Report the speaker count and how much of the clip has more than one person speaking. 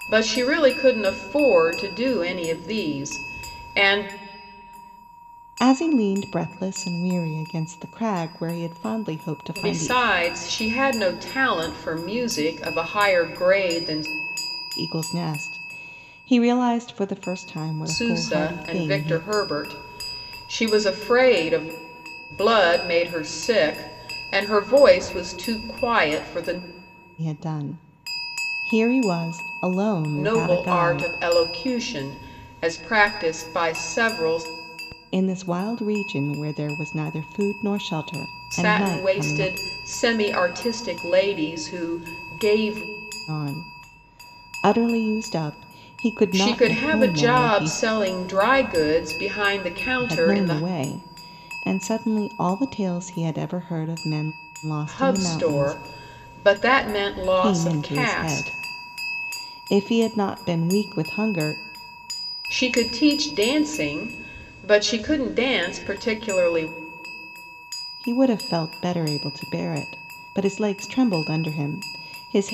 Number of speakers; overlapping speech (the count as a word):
two, about 11%